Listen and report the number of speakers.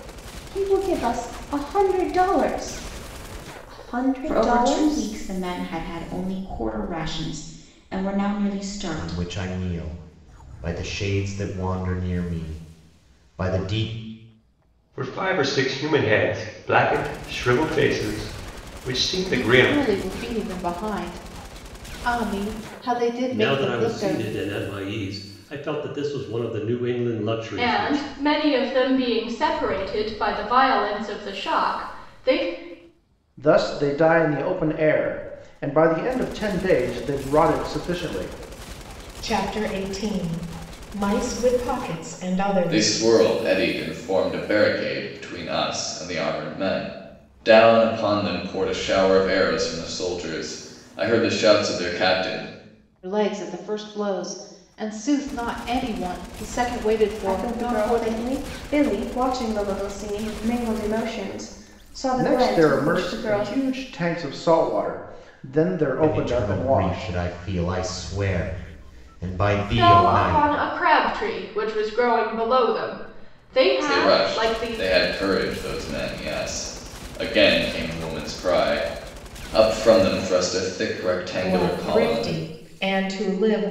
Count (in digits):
10